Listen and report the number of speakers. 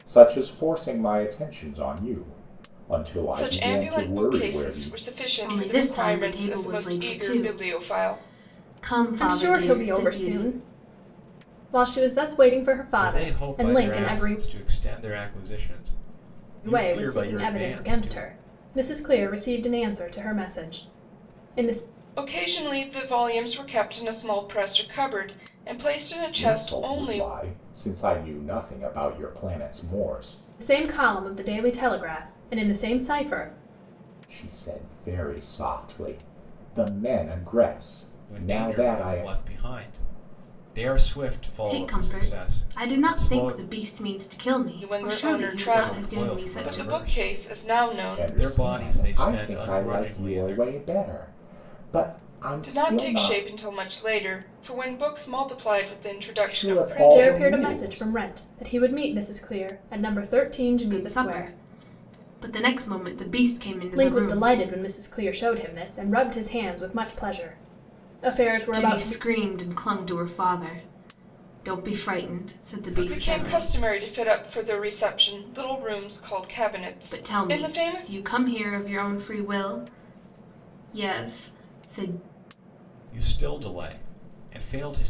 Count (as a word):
five